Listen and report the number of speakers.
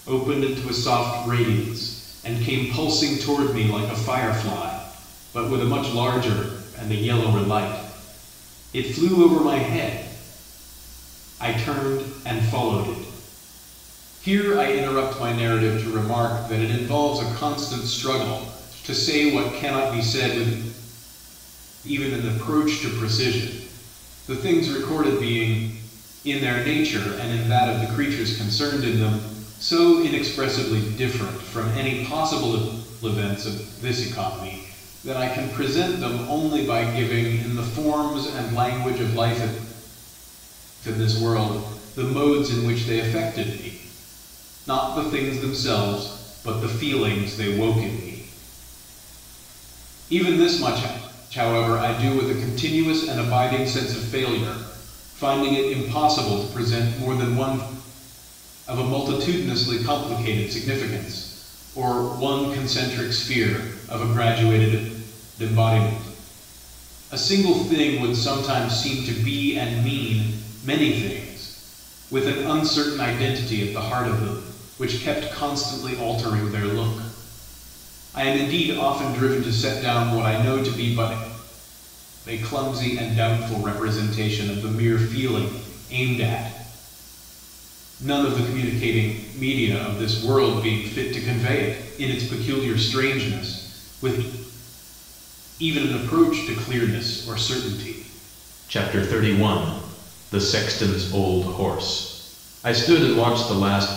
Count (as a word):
one